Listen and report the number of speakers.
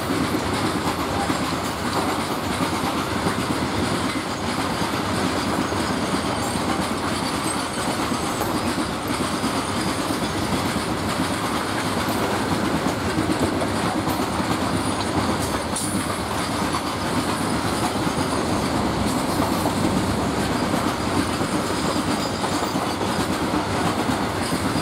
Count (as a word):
zero